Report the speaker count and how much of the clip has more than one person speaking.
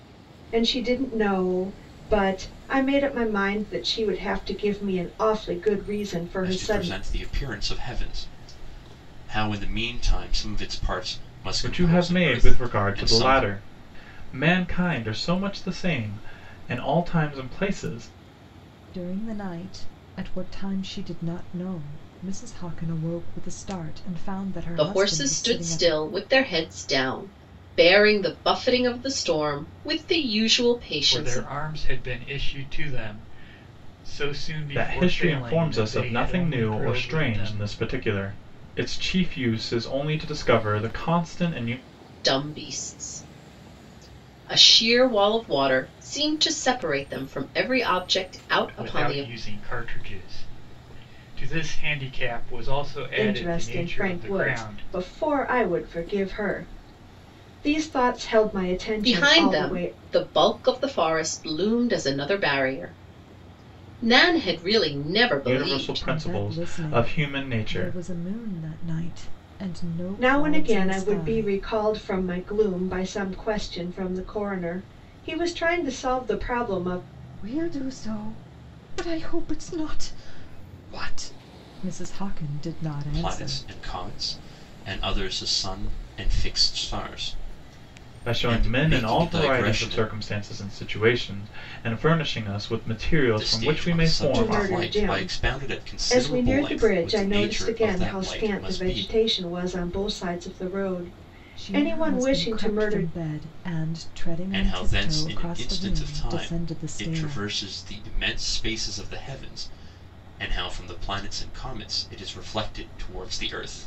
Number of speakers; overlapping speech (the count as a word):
six, about 23%